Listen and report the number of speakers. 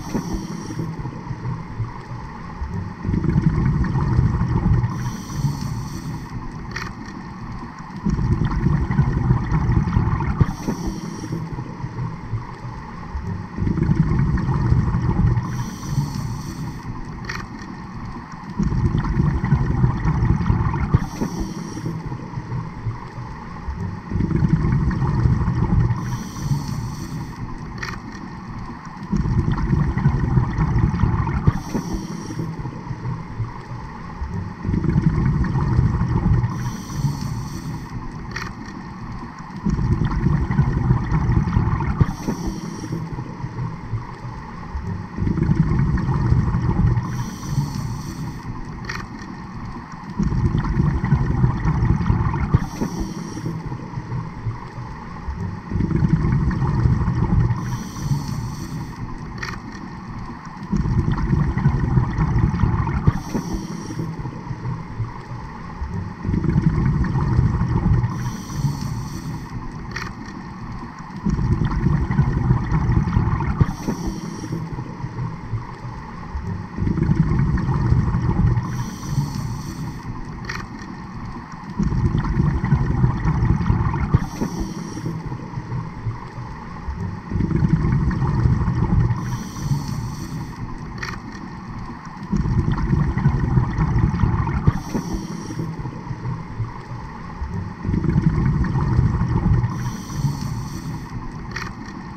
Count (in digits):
0